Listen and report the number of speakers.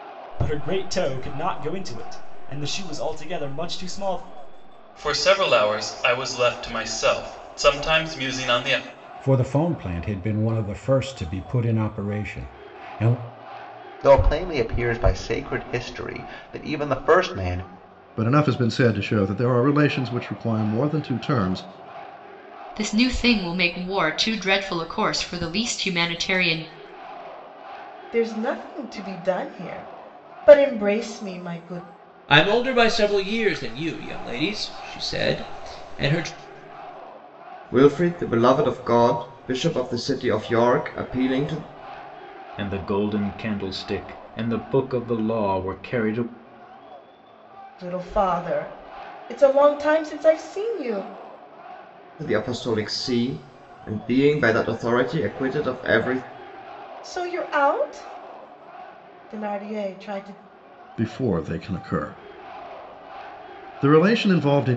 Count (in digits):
10